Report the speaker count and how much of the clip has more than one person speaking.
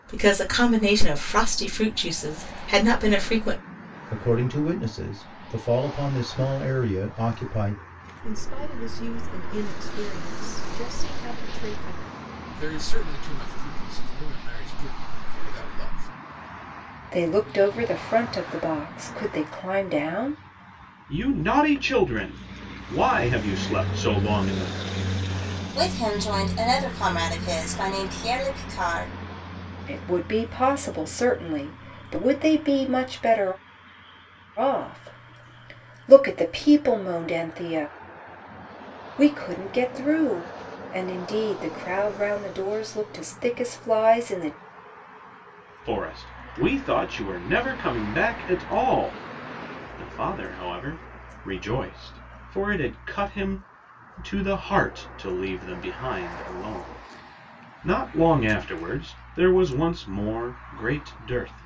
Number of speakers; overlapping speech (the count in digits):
7, no overlap